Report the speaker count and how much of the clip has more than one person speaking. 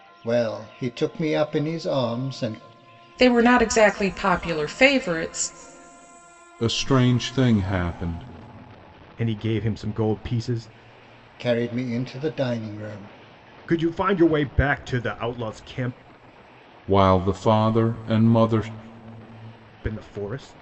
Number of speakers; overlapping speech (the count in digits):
4, no overlap